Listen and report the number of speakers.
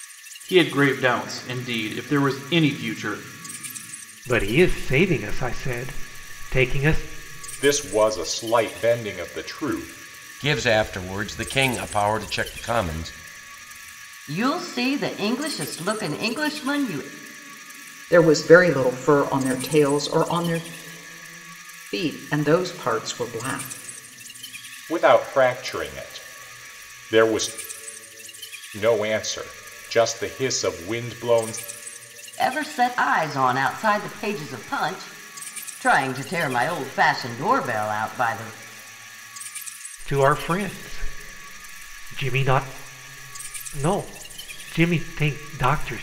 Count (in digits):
6